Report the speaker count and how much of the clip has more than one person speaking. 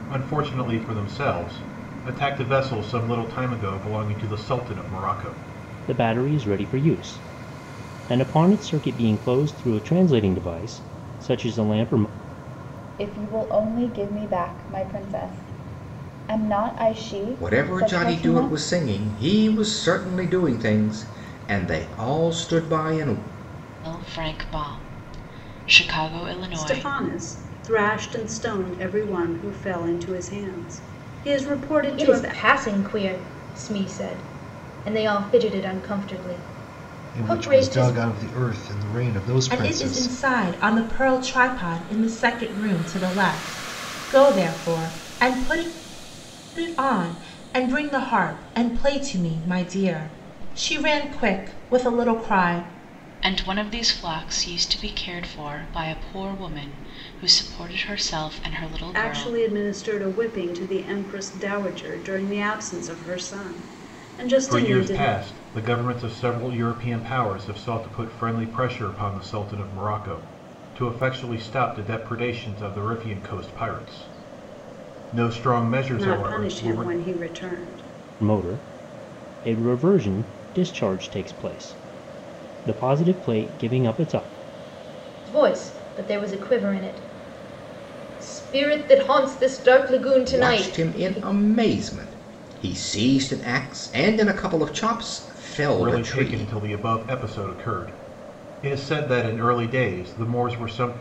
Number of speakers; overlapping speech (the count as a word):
nine, about 7%